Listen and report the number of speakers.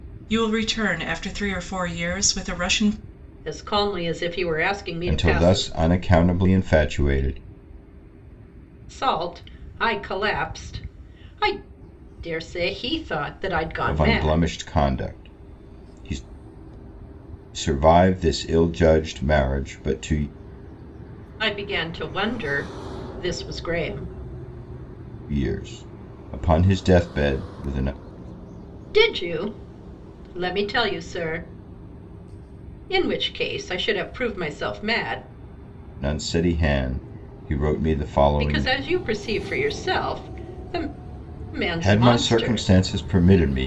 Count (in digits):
3